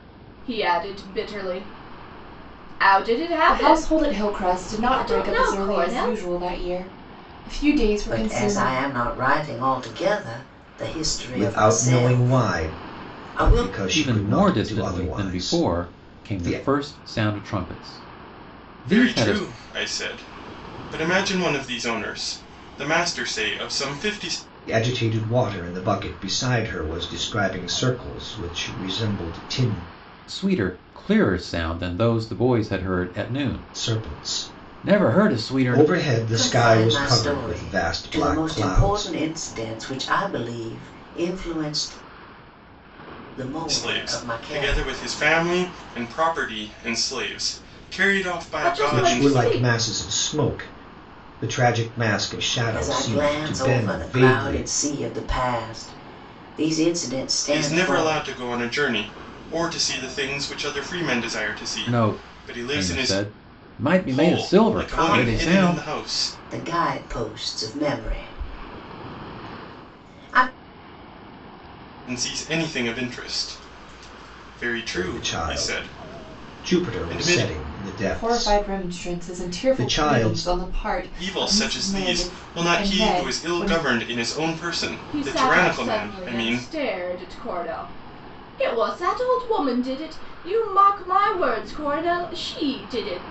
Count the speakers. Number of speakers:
6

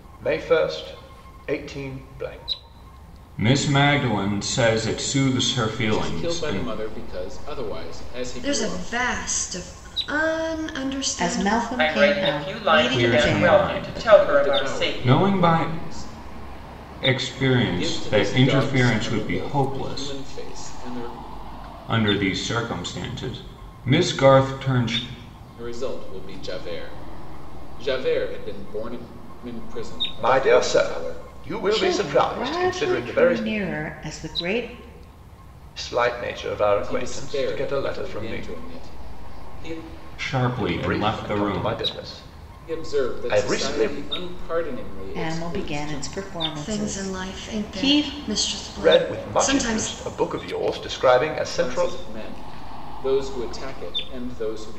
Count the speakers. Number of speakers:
6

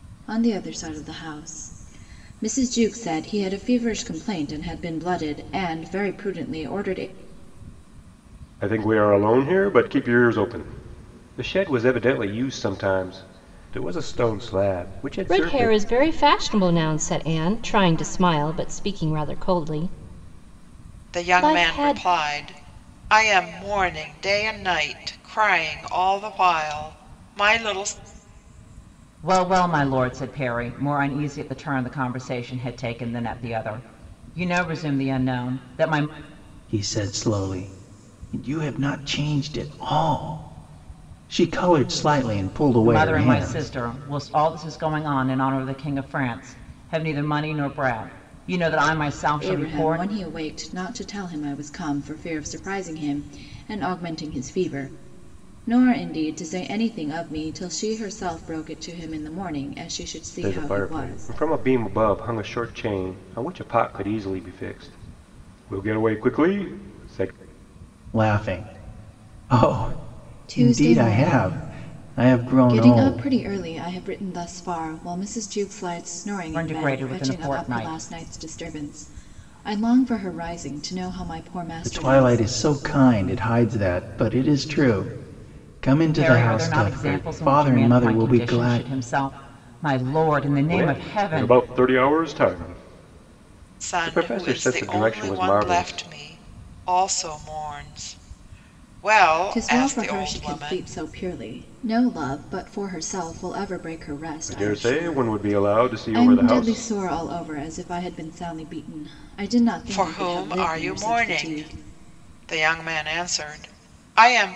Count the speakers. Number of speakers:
6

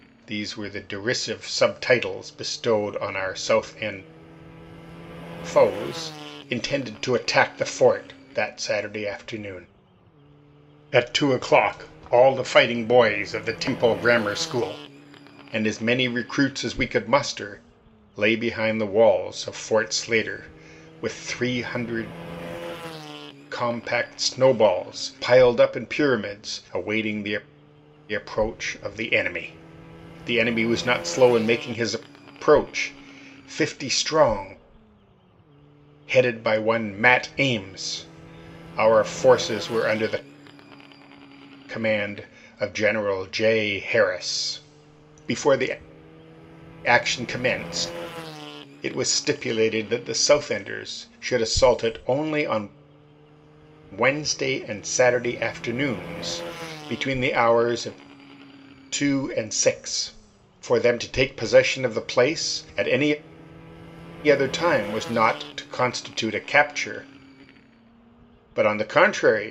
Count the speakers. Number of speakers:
1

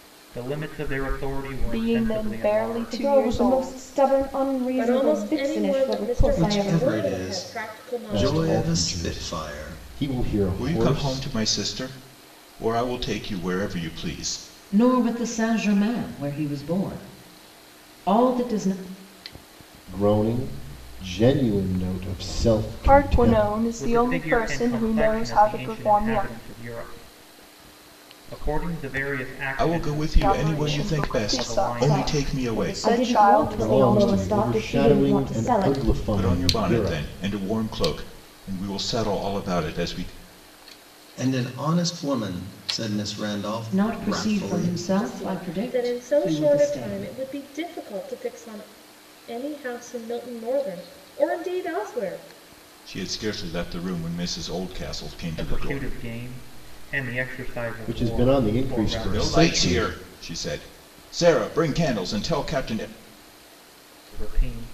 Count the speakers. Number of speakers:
8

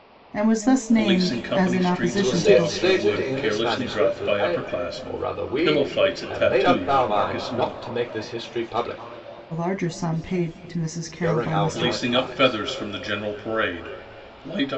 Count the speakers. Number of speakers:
3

